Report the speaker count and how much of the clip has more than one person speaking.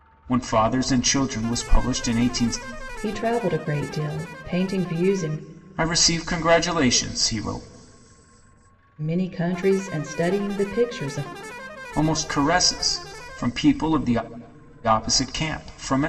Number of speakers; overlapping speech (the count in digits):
2, no overlap